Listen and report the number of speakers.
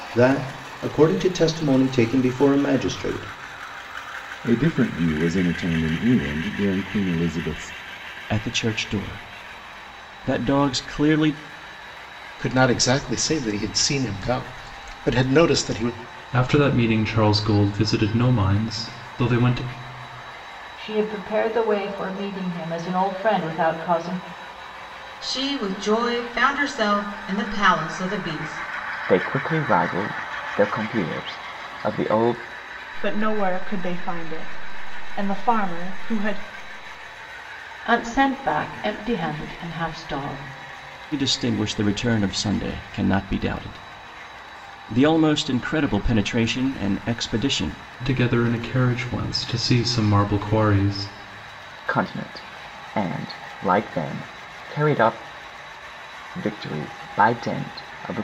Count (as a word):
ten